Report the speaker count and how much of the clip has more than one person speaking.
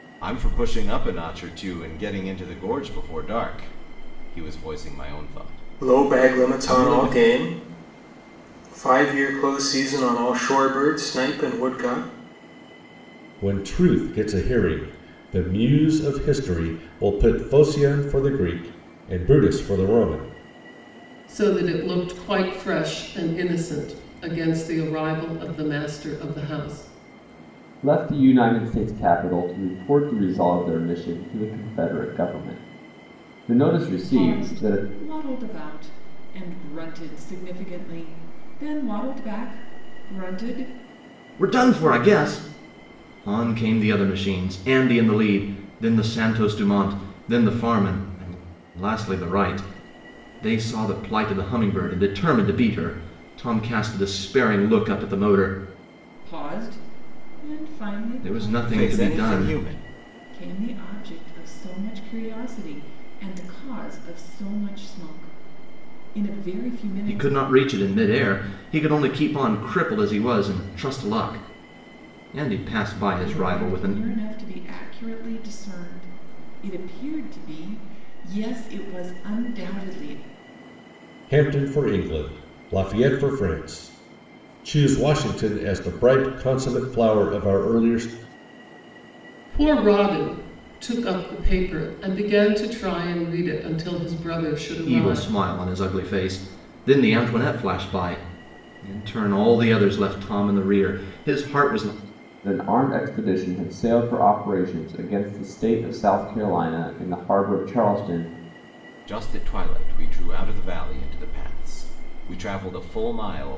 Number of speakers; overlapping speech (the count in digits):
7, about 5%